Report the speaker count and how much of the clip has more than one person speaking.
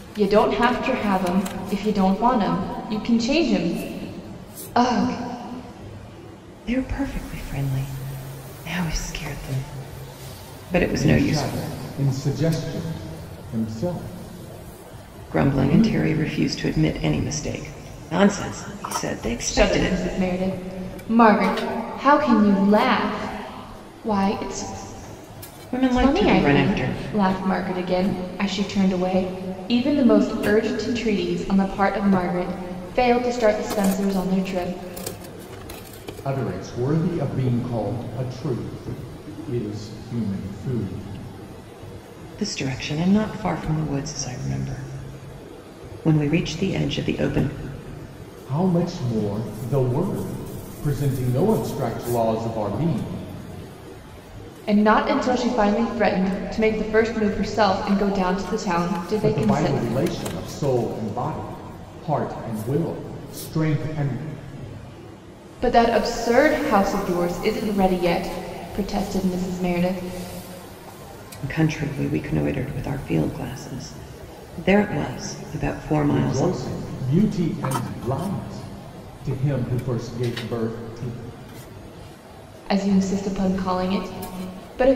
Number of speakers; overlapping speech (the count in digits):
3, about 5%